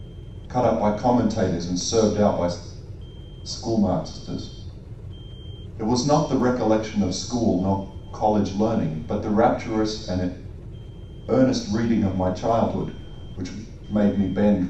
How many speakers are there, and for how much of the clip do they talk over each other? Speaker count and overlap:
one, no overlap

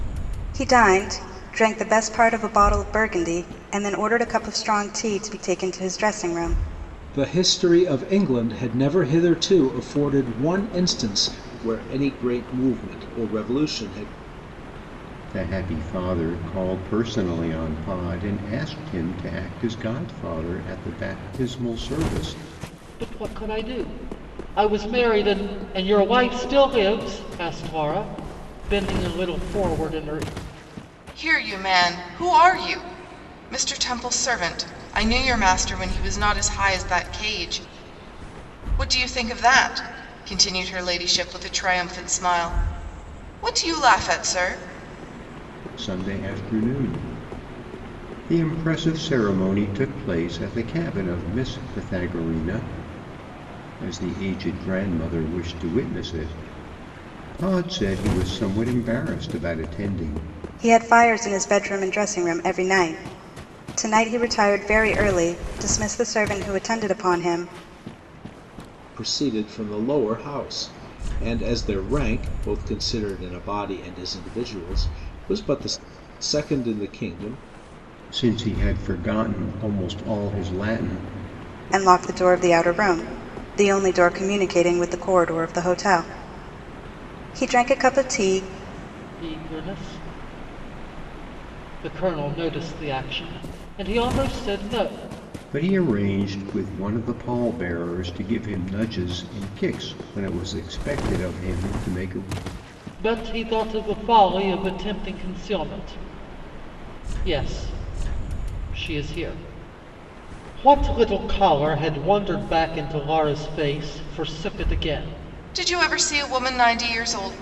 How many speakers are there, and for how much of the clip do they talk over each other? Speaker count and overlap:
five, no overlap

